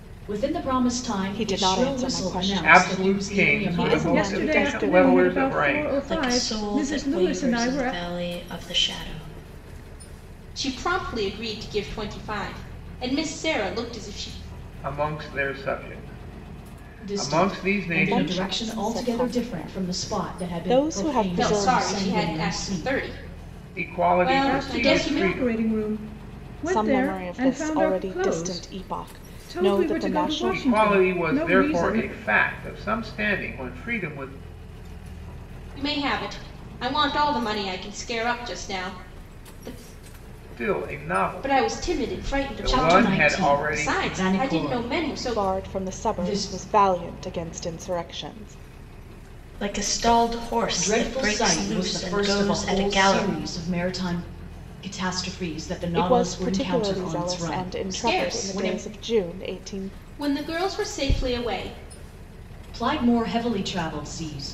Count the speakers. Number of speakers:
six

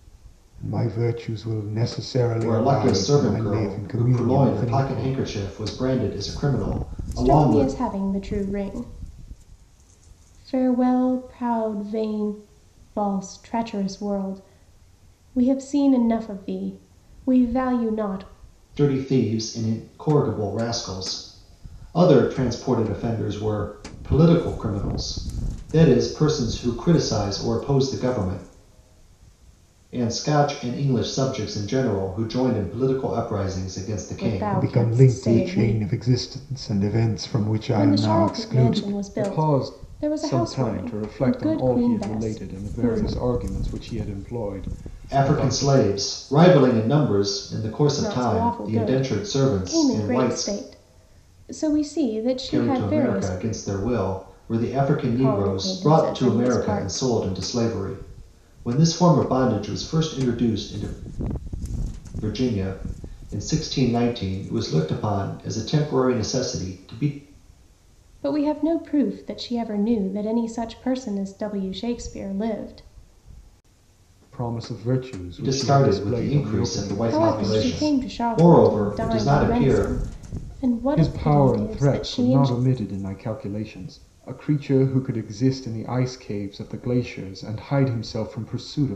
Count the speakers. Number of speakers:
three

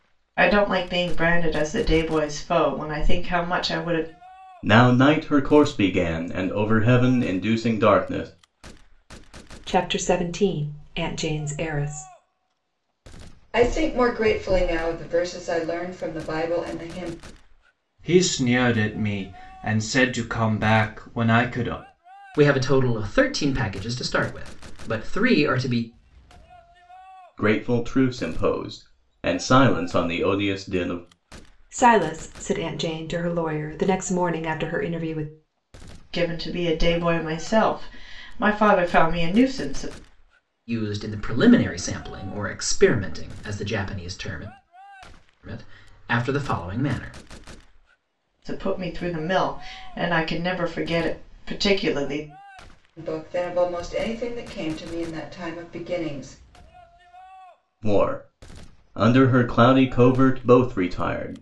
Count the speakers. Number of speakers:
six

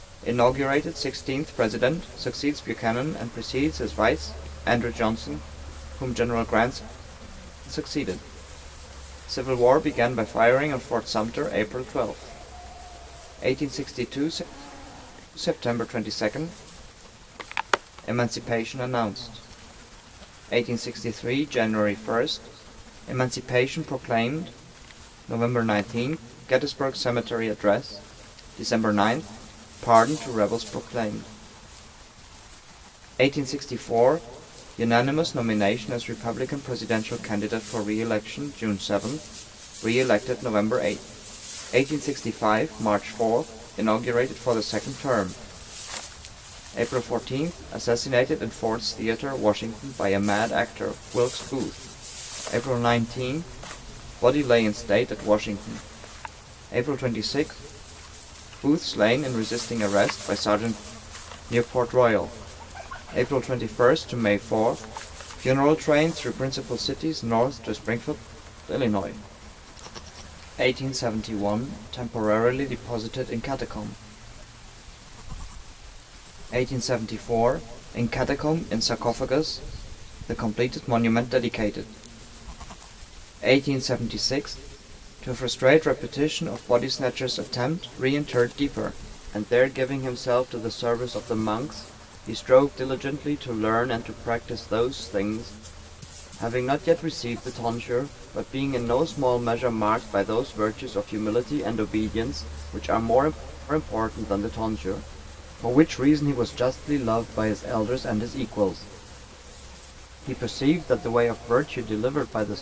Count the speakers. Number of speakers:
one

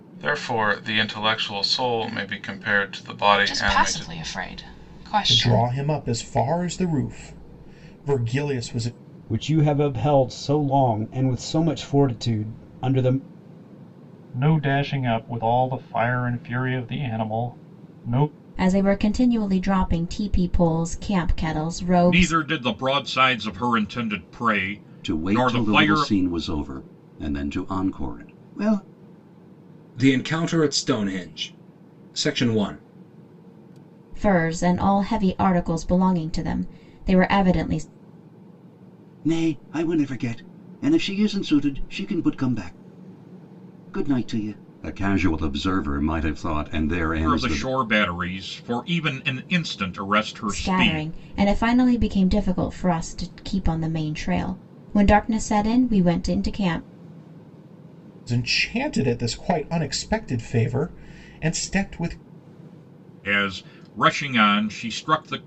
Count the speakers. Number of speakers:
nine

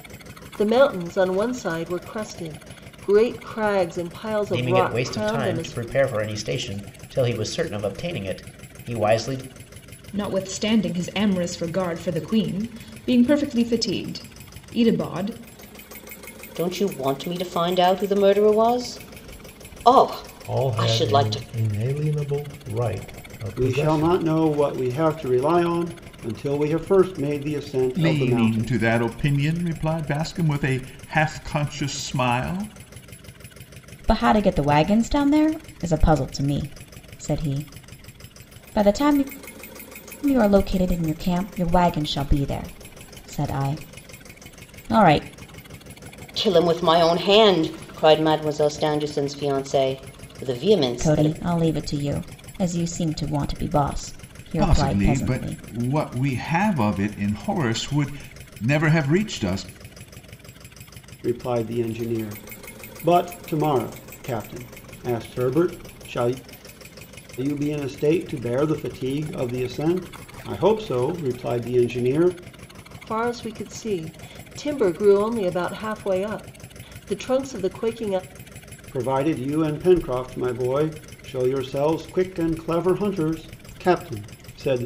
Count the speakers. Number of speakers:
eight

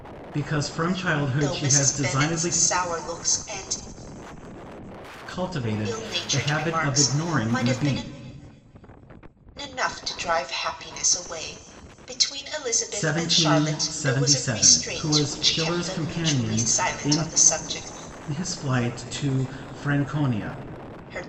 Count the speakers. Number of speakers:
two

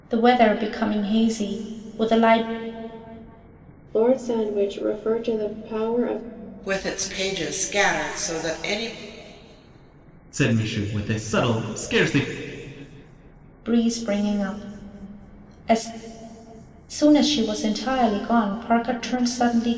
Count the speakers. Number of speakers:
four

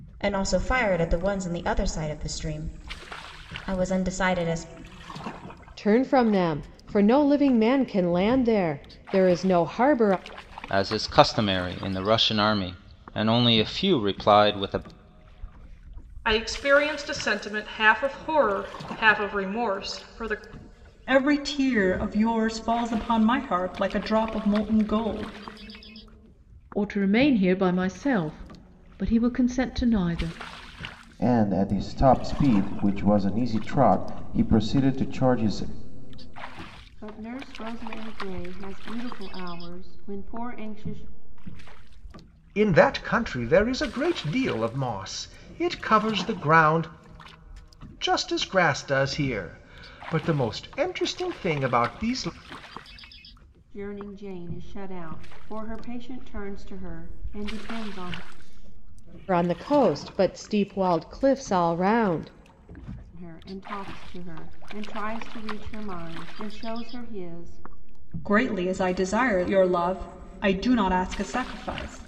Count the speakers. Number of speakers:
nine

